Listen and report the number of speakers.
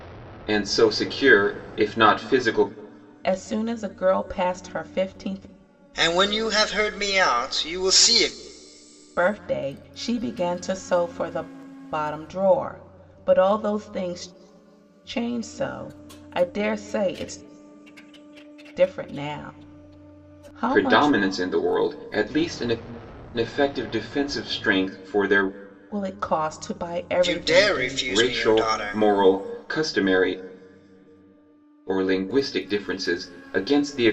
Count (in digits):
3